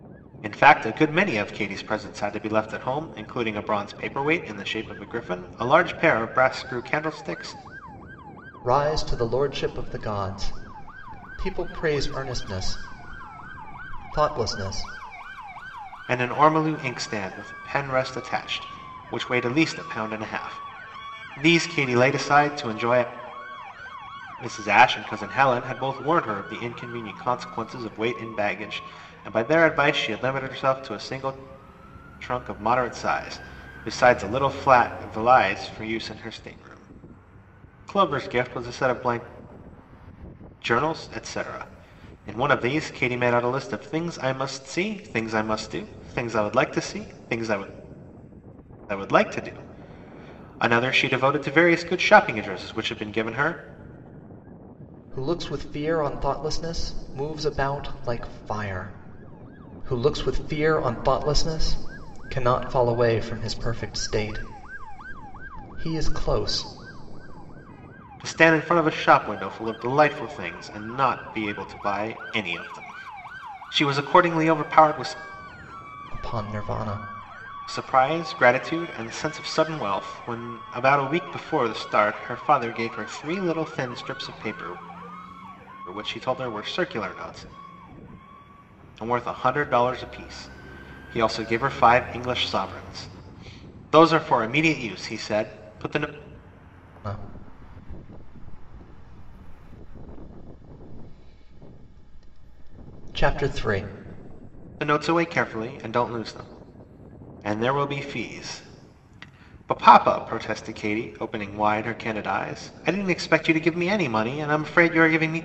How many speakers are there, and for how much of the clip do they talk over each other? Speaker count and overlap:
2, no overlap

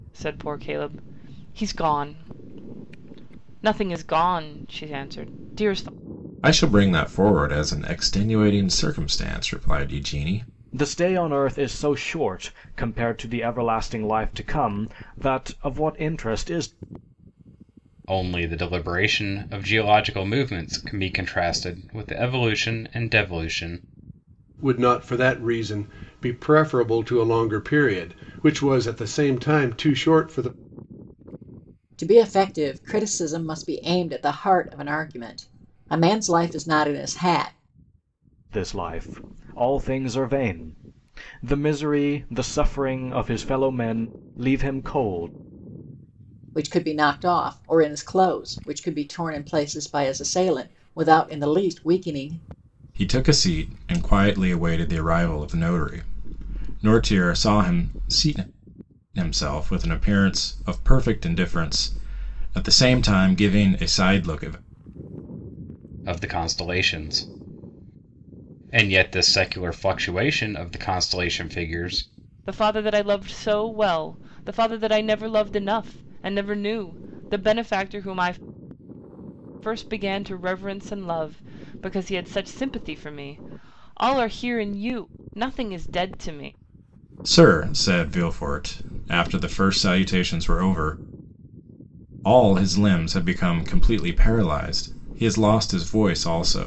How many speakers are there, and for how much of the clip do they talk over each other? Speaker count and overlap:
6, no overlap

